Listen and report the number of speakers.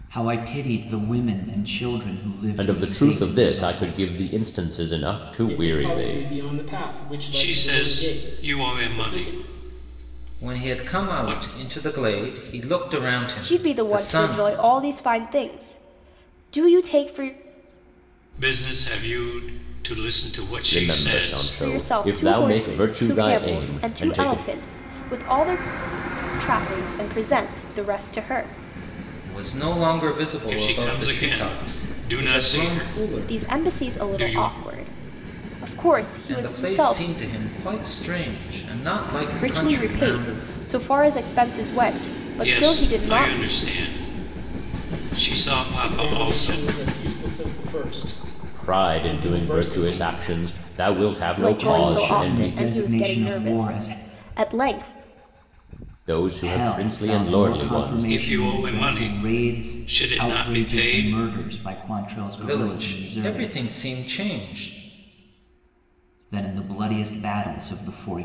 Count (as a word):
six